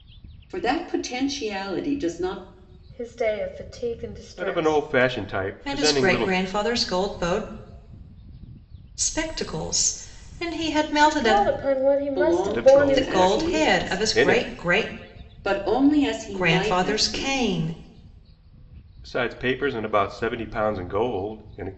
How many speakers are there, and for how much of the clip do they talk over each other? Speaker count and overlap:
four, about 25%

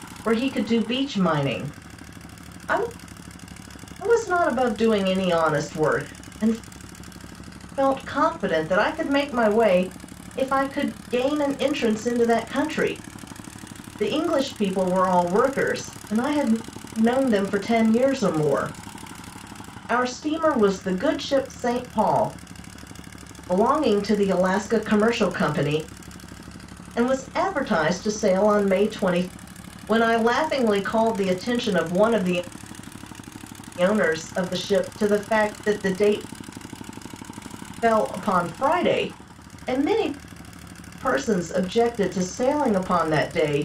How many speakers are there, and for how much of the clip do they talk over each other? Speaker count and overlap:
one, no overlap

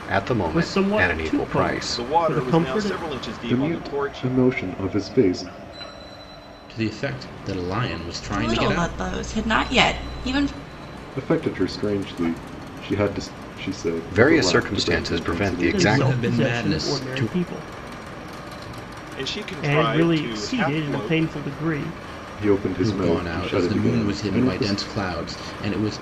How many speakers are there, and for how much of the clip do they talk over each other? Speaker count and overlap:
six, about 42%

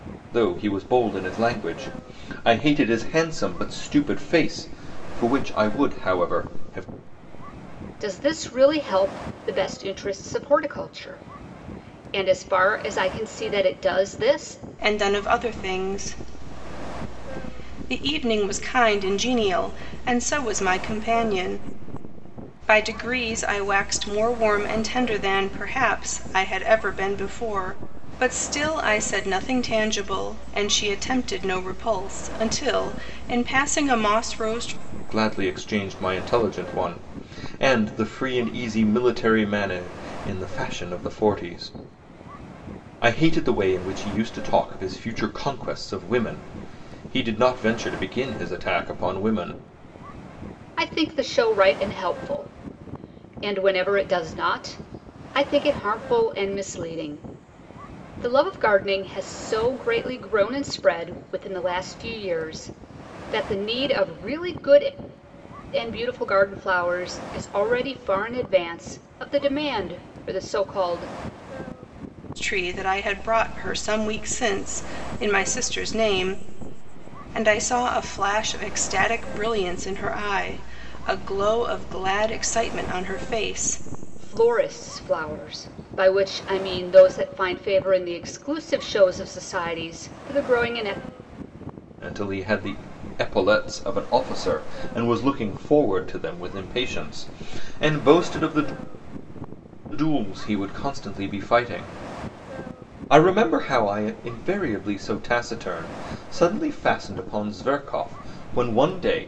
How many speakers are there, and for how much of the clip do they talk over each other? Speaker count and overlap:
three, no overlap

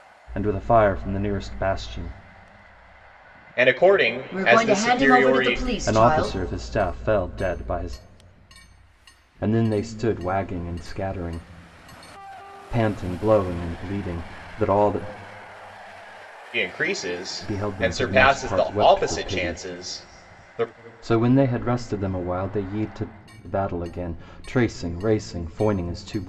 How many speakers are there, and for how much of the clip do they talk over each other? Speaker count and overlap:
three, about 15%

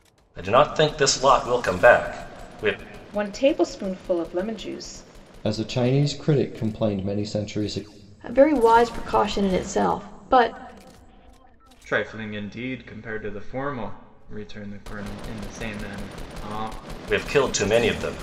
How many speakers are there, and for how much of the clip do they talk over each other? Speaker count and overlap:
five, no overlap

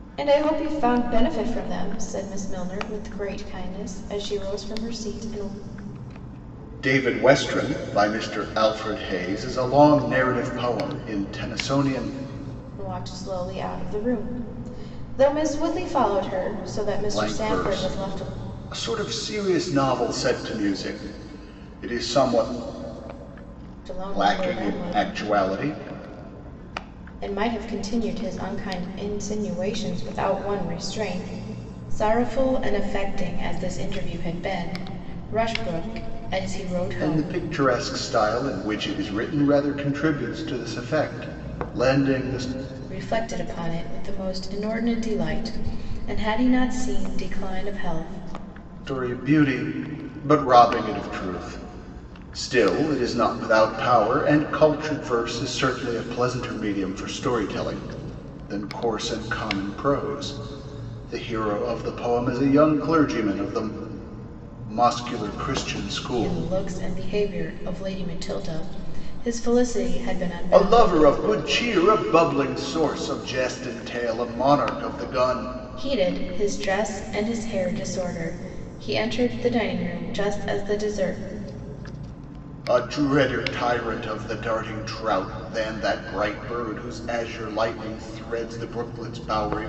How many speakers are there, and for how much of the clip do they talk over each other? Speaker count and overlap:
two, about 4%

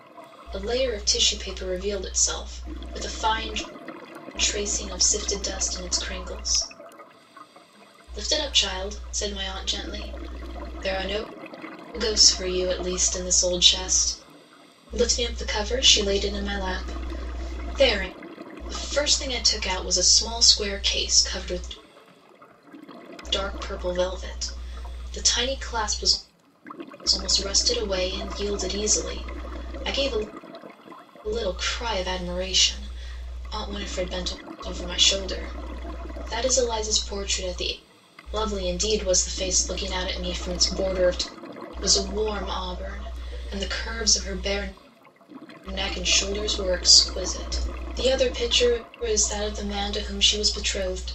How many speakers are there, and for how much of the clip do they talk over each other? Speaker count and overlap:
one, no overlap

